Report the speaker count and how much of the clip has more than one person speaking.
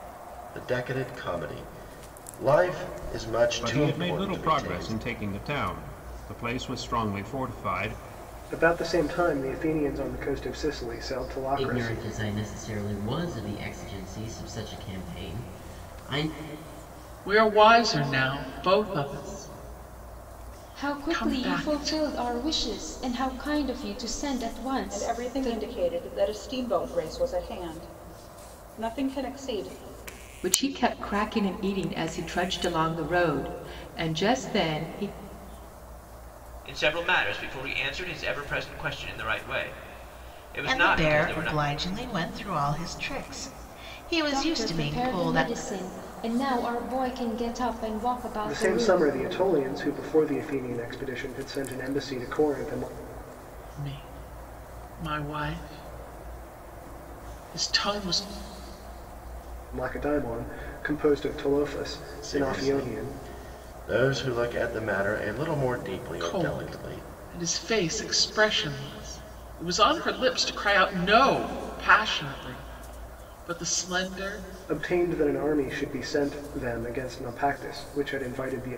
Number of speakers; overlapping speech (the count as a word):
ten, about 11%